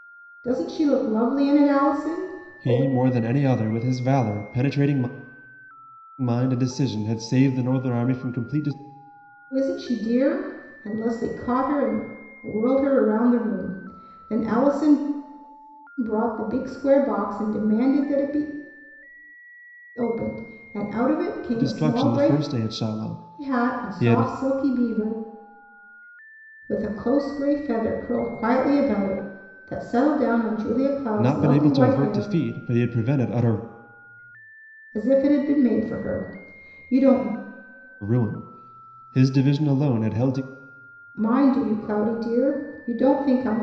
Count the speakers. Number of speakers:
two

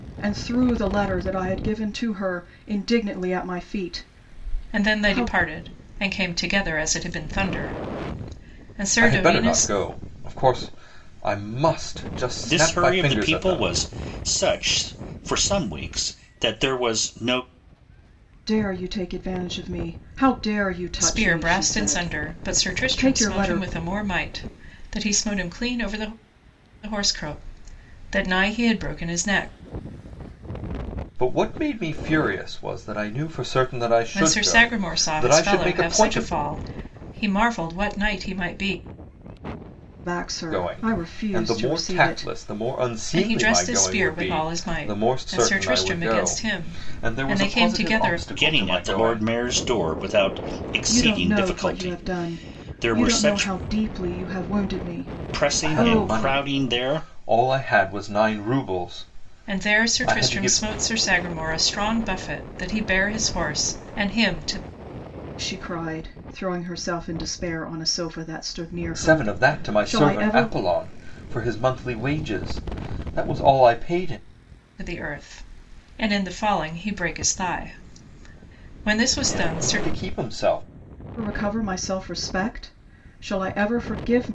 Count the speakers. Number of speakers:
four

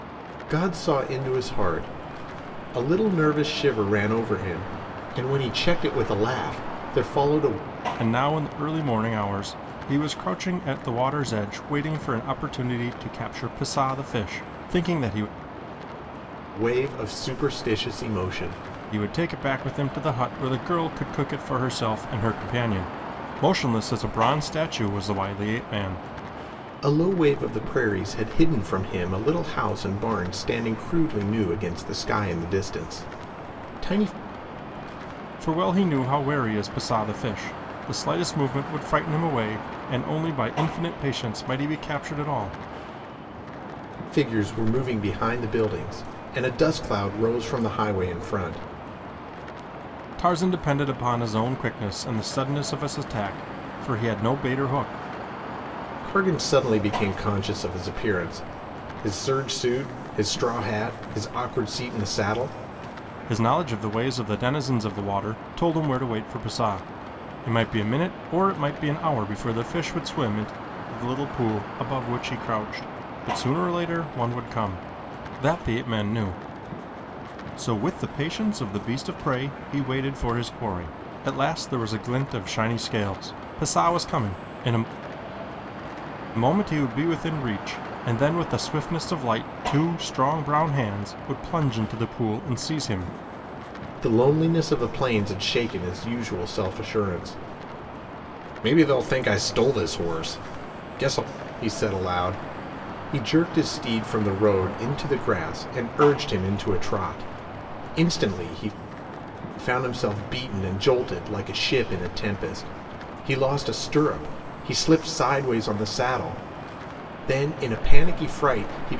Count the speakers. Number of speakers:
two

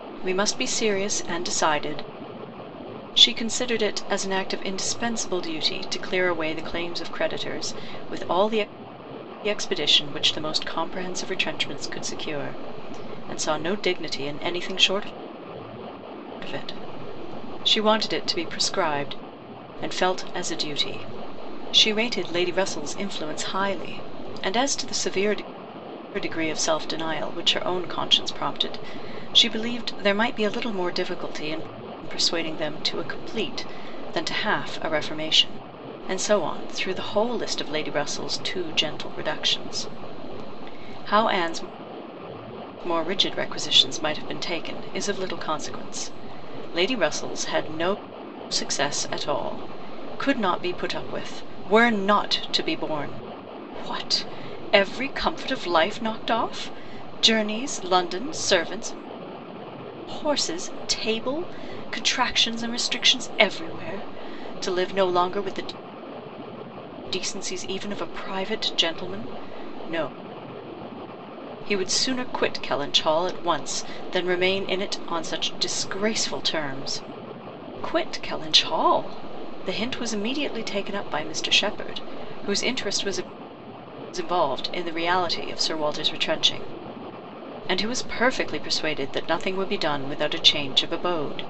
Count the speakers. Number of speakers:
one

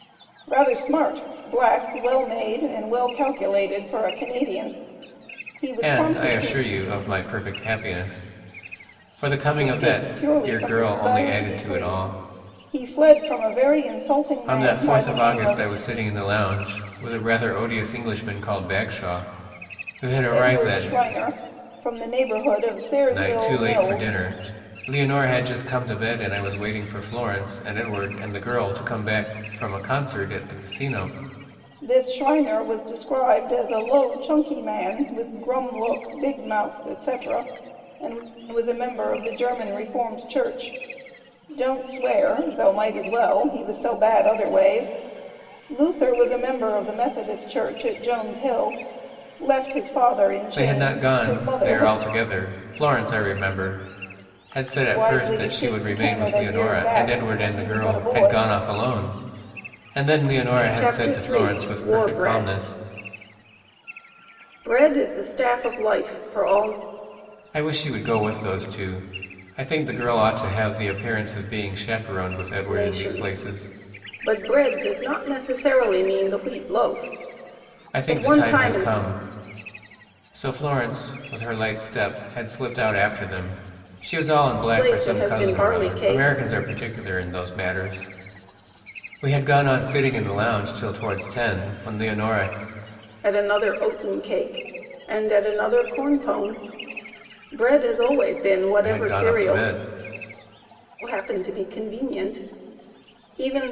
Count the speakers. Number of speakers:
two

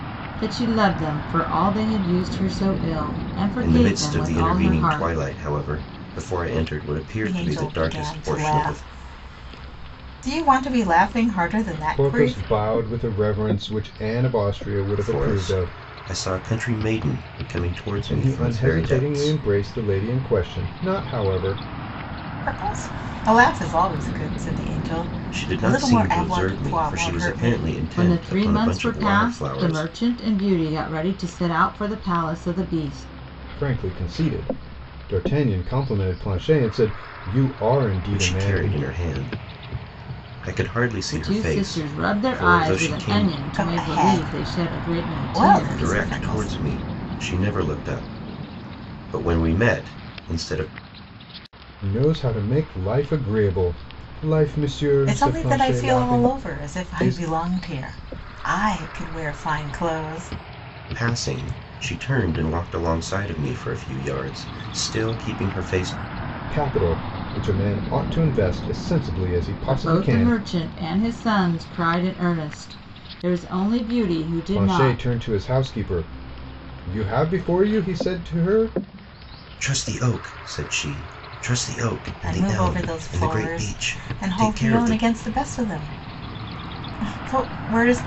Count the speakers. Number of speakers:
four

